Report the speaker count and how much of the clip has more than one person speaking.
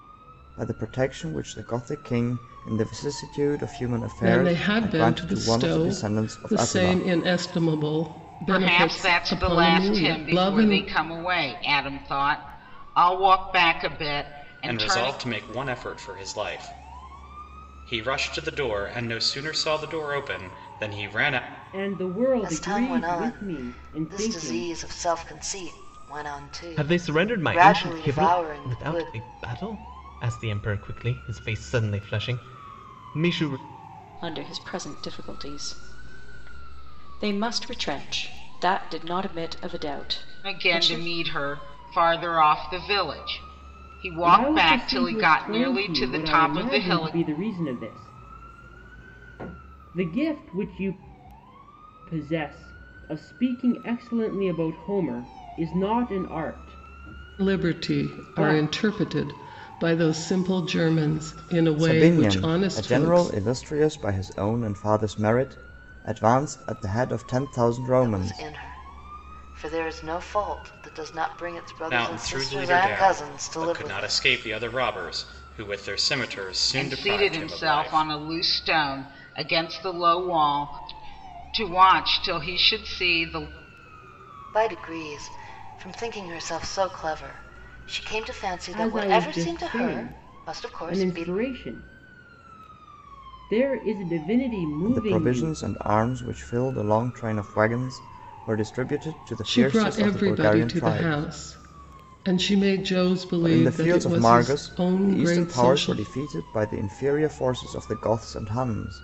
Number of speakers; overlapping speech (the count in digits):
8, about 27%